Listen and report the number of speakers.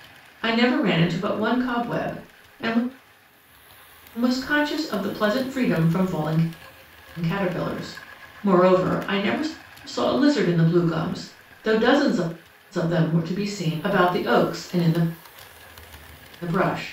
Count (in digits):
1